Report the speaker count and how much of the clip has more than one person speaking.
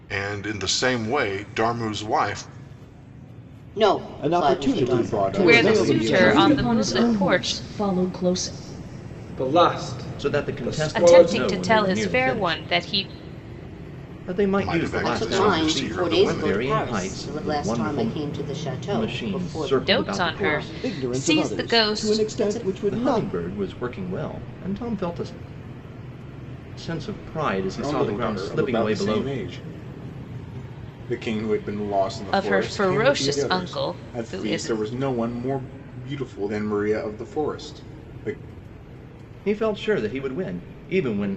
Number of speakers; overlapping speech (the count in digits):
8, about 43%